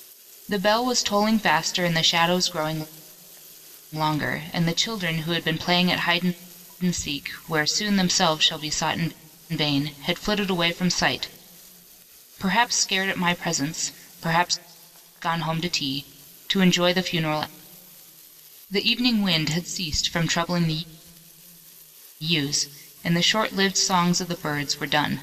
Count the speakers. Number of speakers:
1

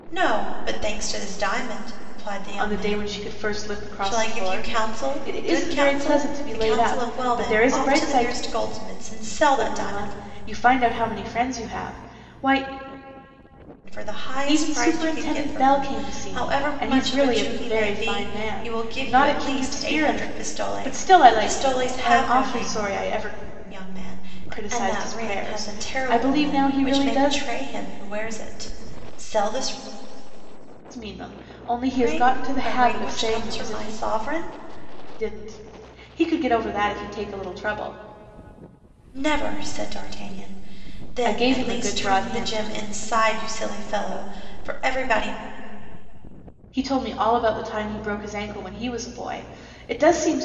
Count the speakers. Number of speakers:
2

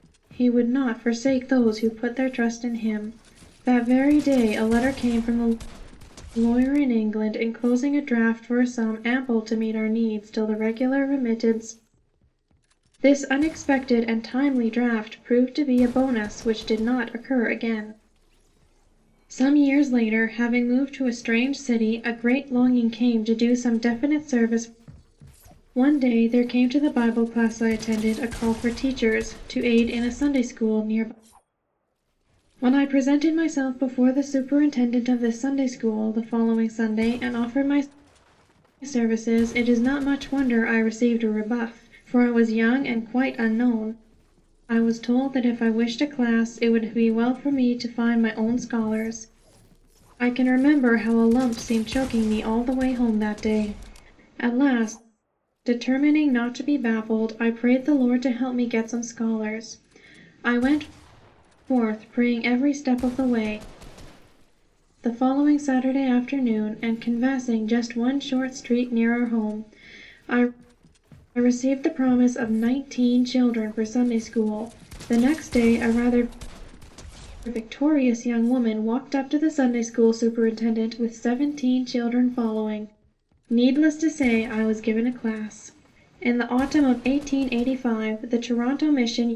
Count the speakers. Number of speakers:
1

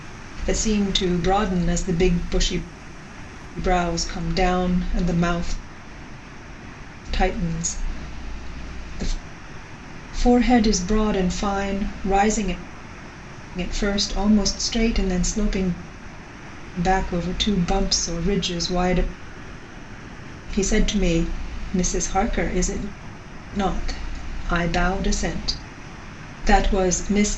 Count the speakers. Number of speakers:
1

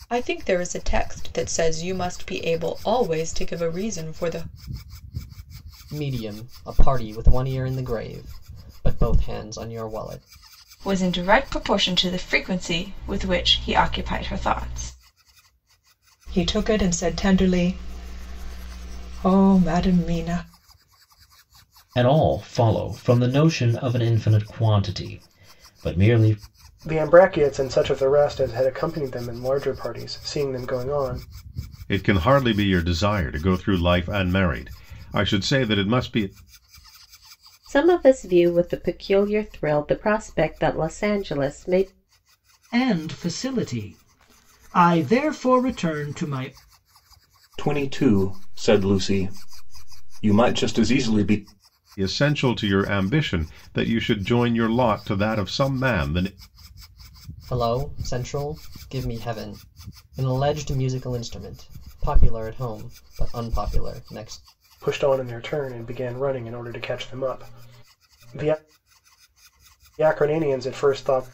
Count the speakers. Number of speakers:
10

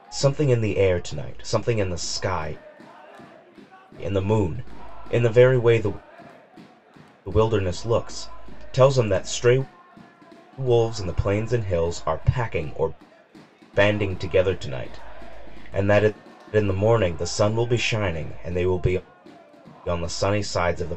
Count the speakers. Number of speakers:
1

